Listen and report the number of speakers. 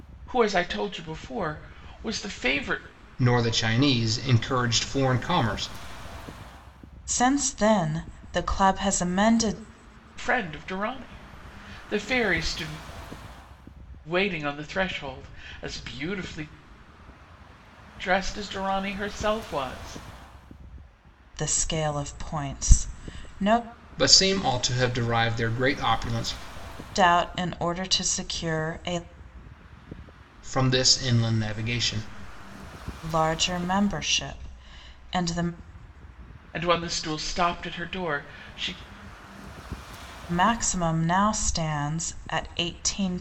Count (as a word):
three